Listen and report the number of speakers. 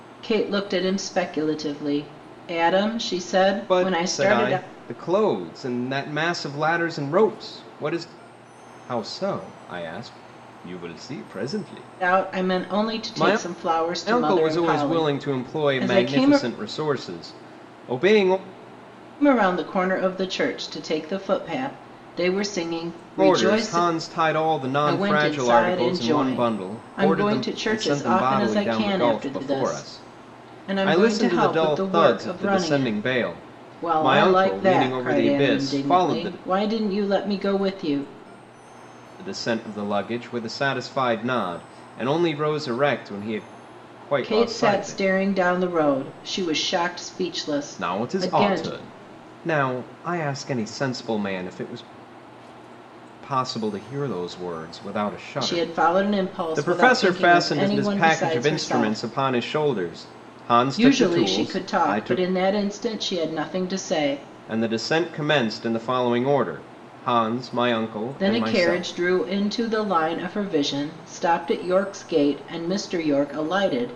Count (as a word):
two